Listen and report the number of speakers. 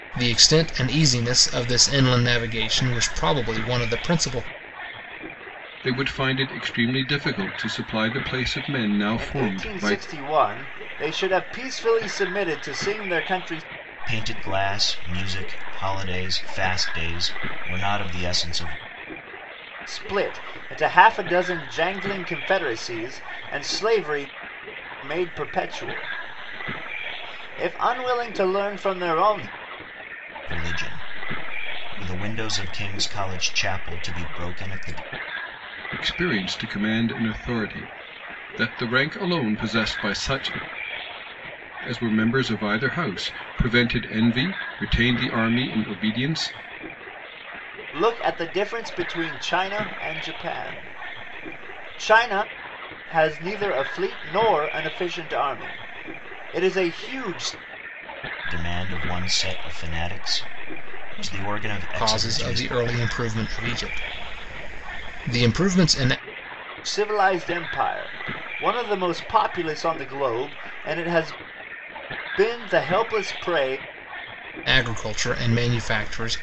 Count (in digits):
4